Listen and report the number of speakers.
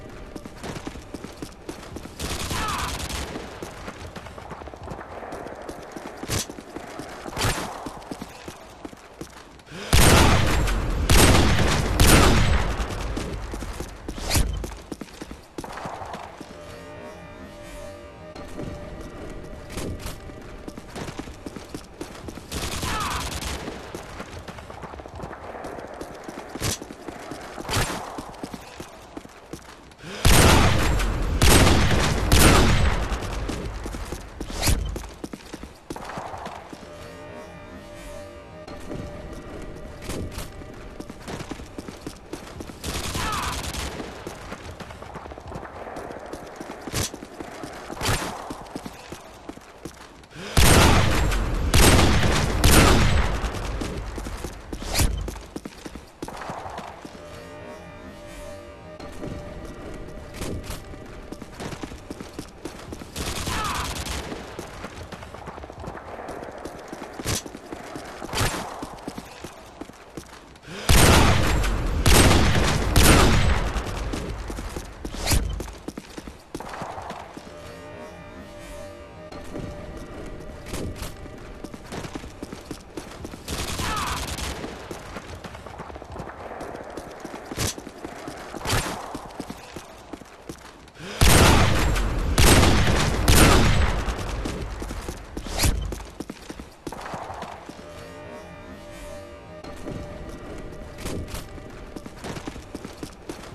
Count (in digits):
0